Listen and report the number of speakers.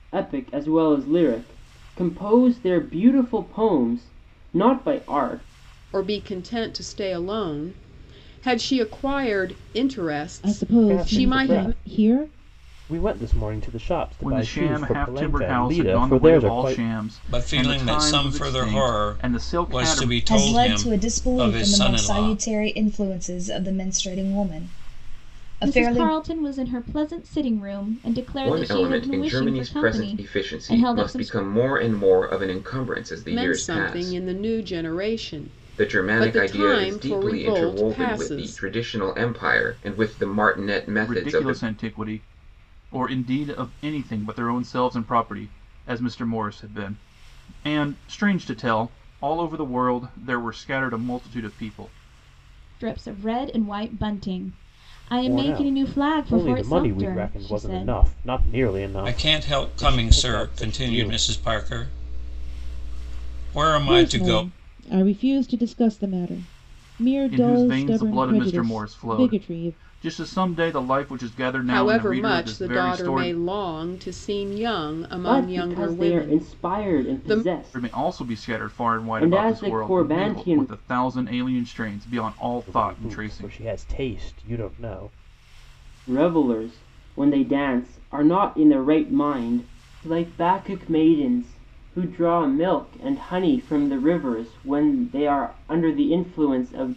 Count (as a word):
nine